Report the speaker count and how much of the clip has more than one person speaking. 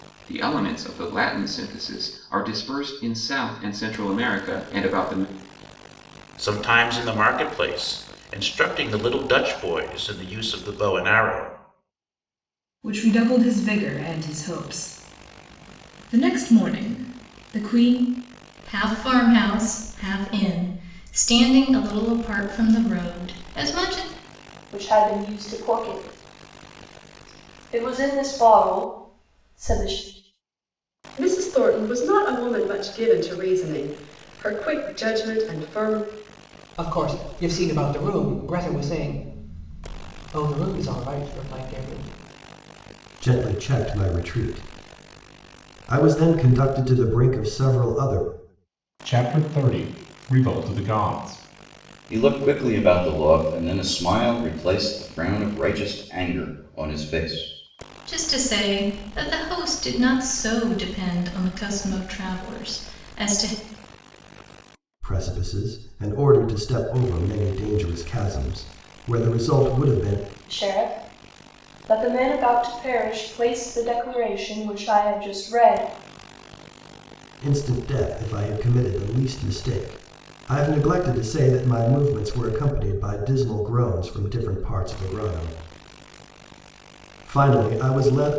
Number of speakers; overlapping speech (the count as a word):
ten, no overlap